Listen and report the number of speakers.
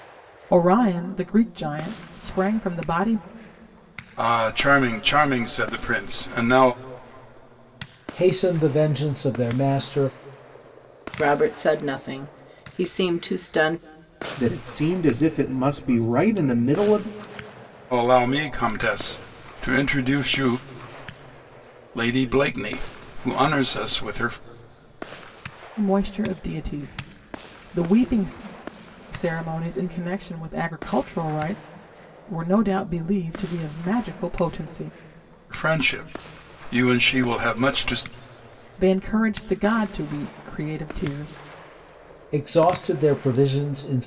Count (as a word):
five